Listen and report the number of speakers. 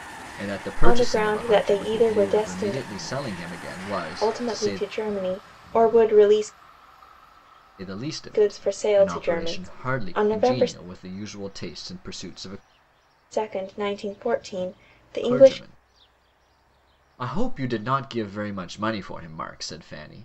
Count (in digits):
2